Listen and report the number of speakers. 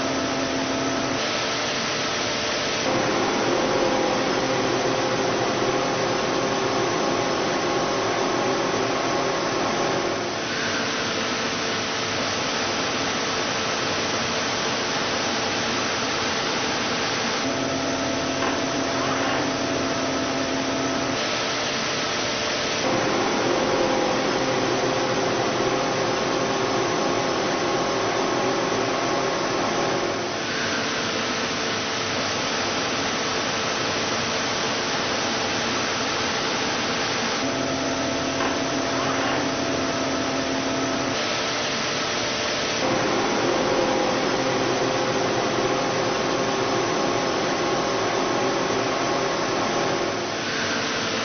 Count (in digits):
0